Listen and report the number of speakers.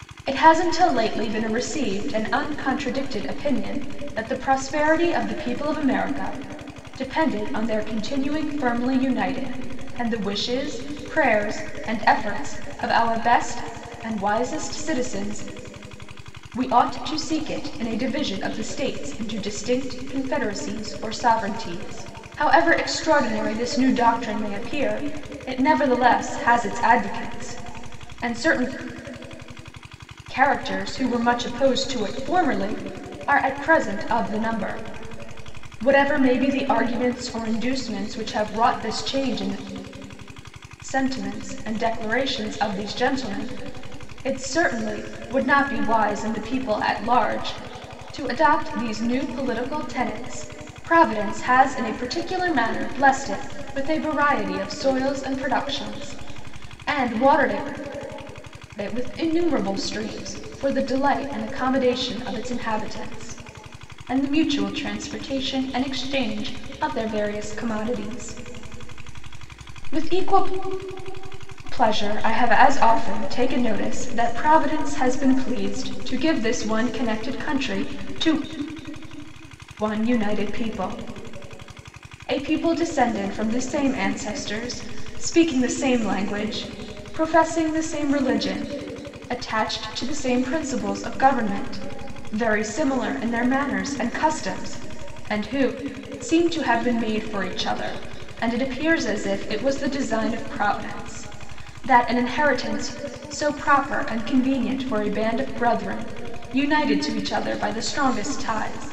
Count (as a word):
one